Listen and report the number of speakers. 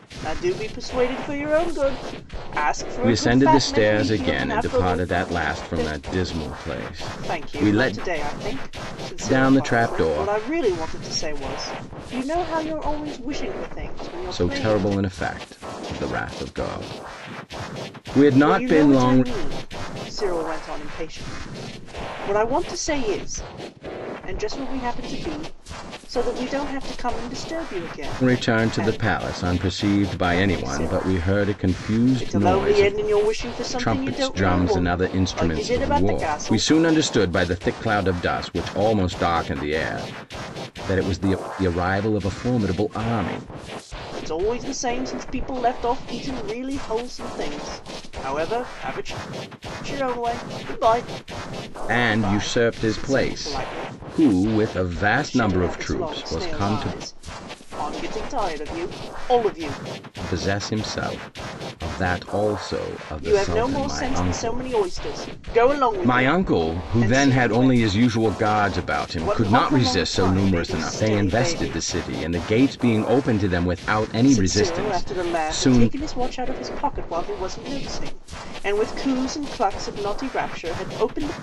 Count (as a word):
two